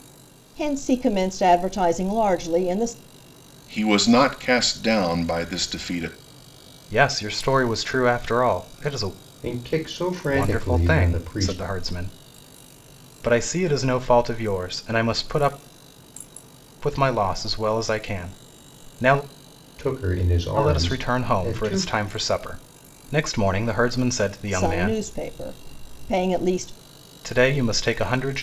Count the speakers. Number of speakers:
4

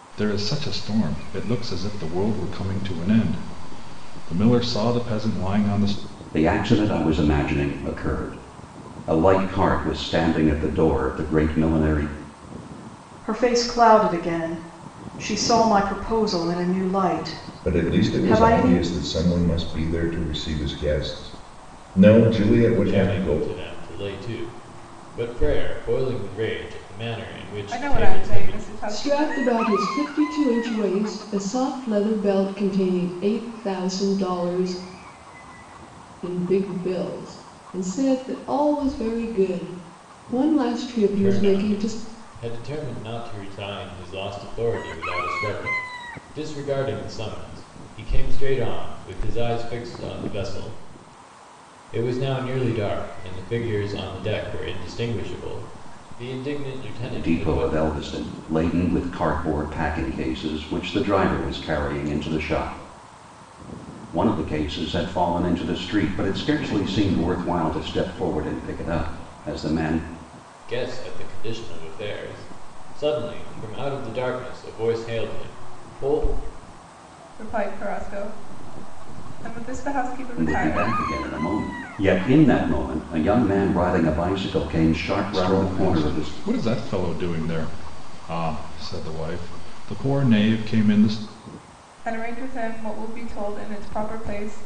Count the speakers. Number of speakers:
7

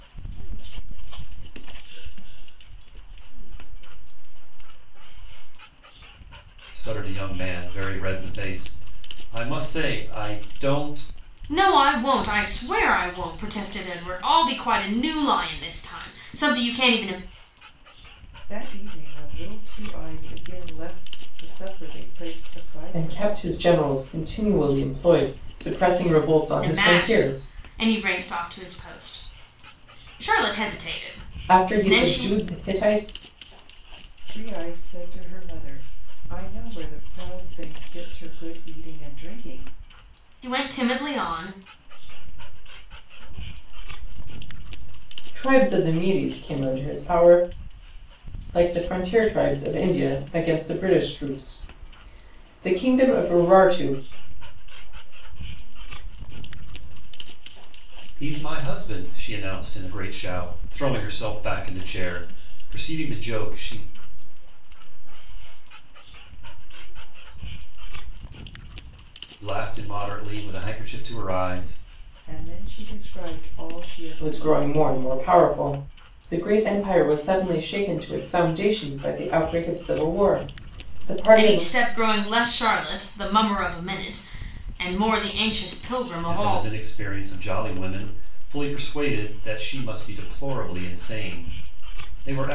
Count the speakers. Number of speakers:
5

